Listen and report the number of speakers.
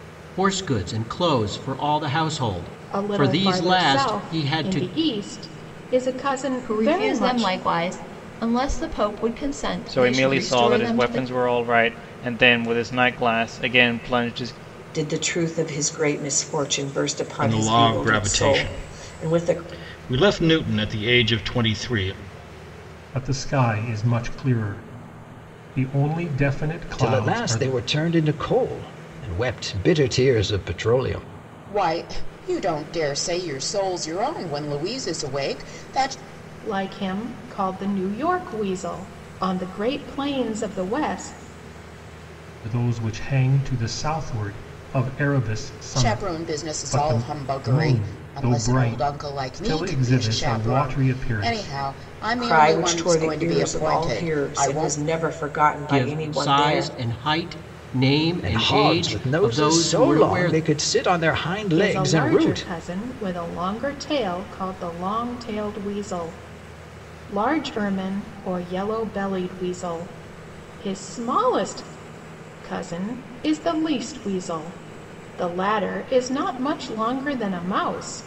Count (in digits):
9